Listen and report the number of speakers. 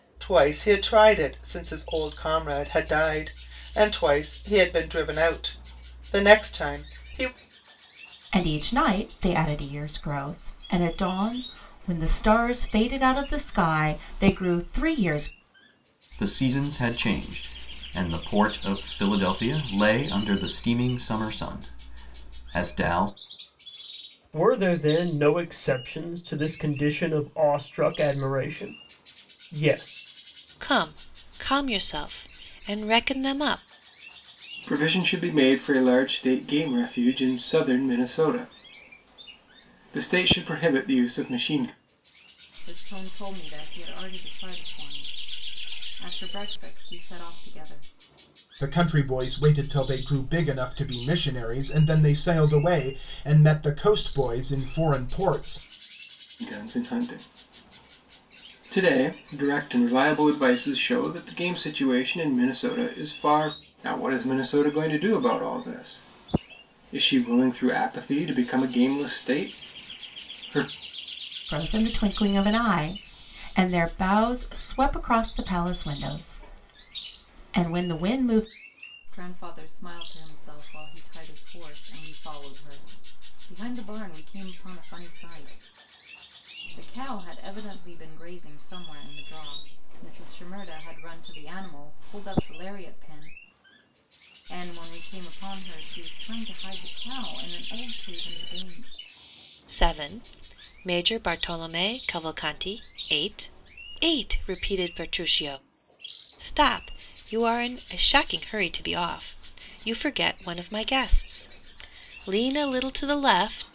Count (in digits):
8